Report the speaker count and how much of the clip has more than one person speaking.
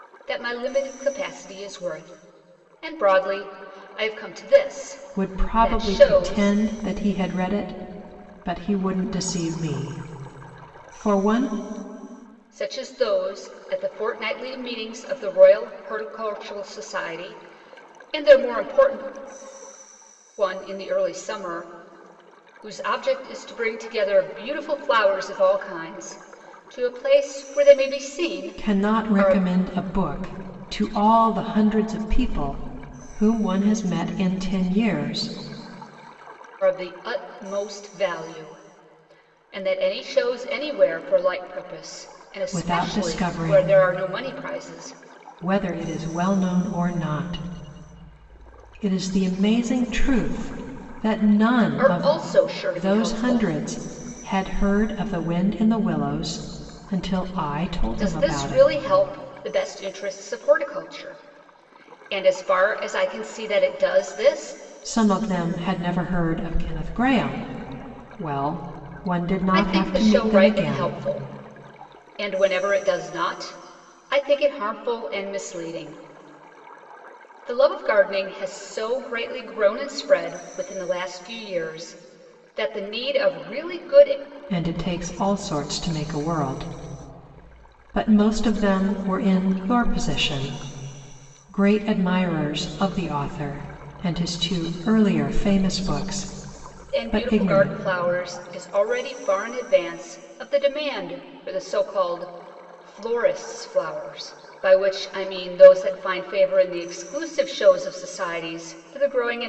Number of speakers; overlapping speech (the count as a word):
two, about 7%